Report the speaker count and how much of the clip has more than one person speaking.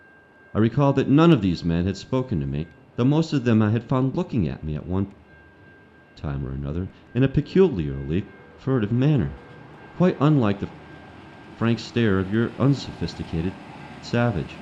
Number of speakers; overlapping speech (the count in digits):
1, no overlap